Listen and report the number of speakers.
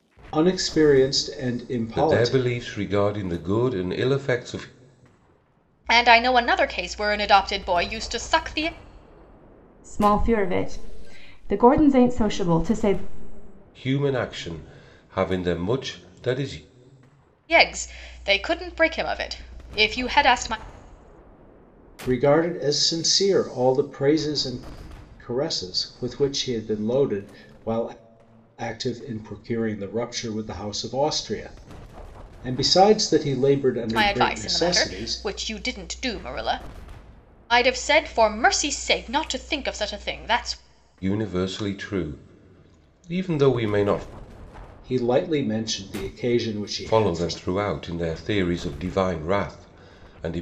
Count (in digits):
4